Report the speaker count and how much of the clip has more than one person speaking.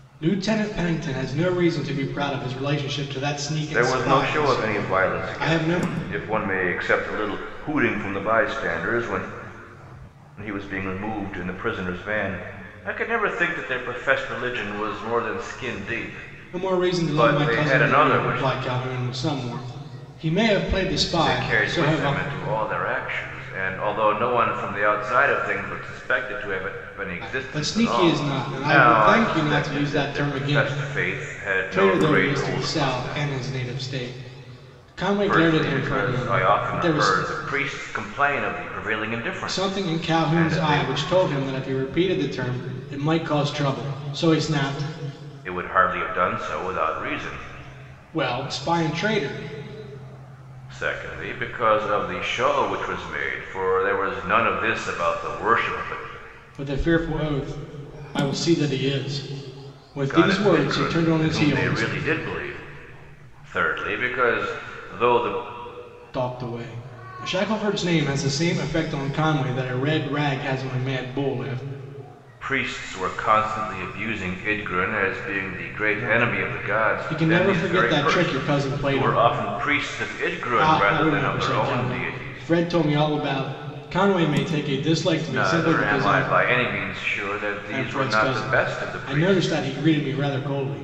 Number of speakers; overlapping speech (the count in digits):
2, about 26%